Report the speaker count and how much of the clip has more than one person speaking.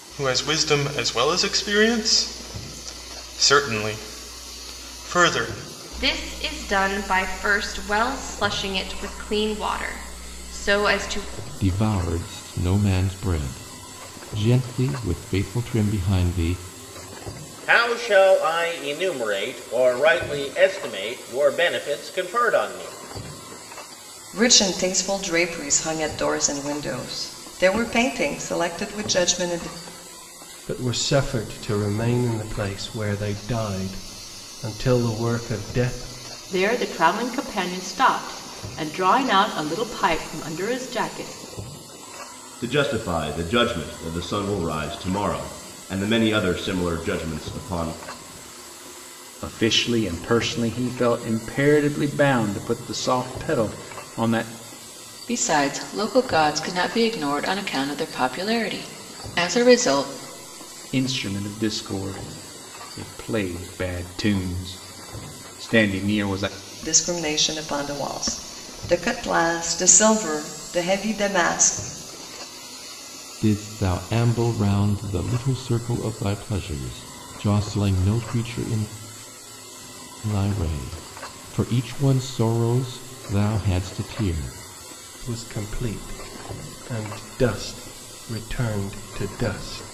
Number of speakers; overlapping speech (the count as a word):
ten, no overlap